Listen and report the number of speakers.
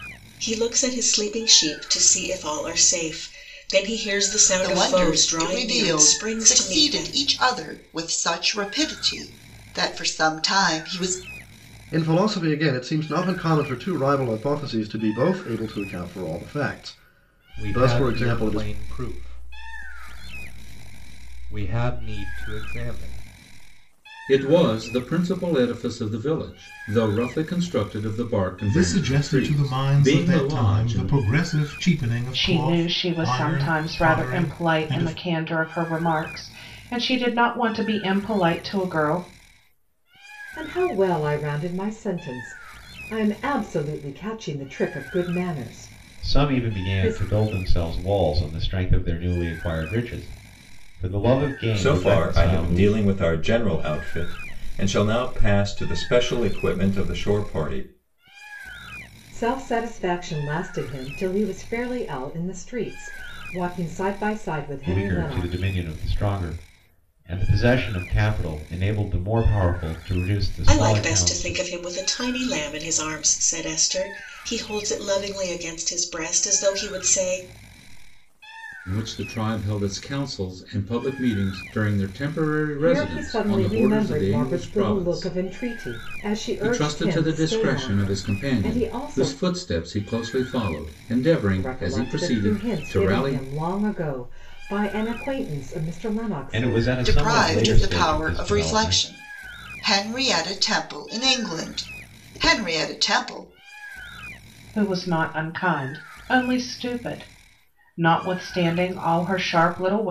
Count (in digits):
10